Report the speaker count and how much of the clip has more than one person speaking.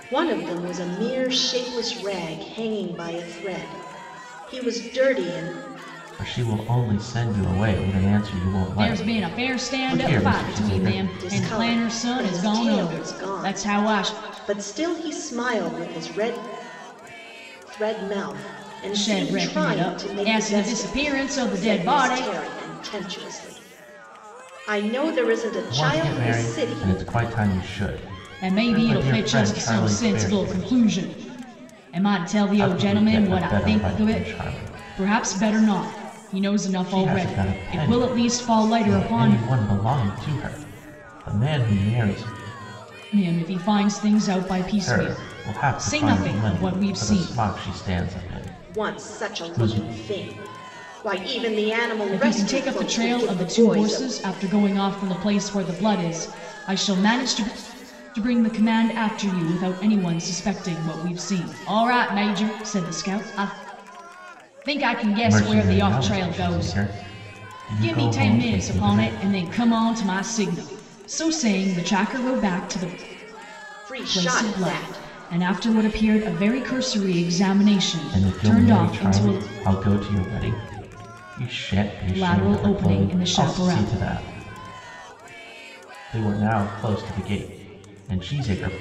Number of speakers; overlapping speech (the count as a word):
three, about 34%